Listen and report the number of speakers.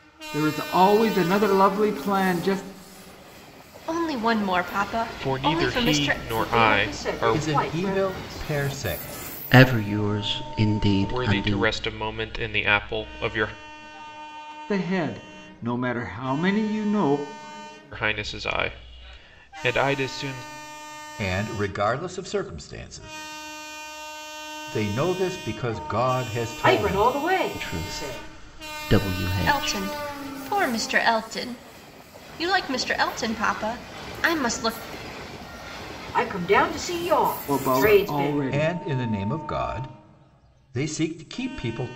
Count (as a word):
six